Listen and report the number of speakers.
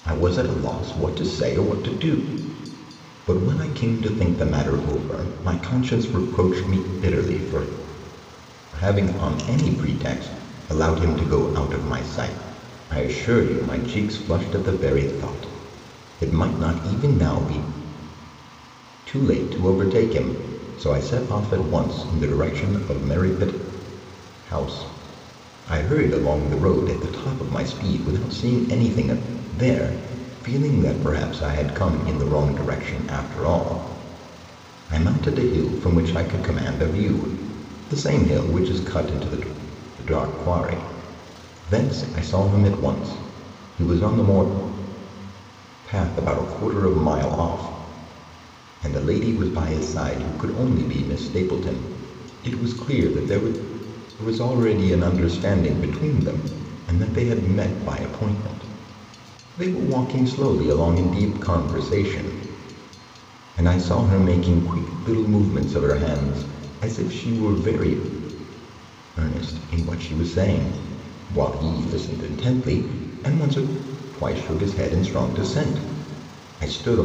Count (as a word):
one